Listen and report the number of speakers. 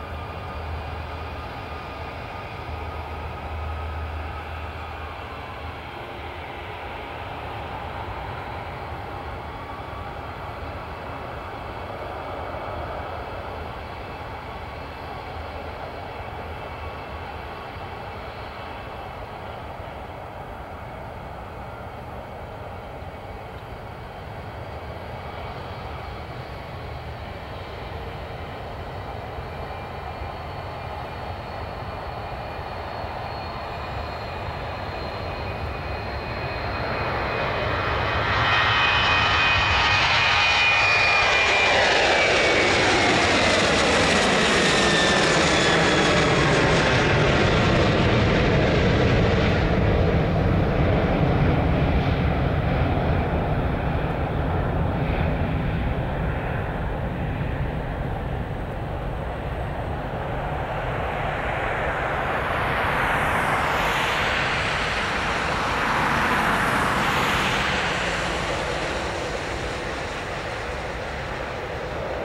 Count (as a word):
zero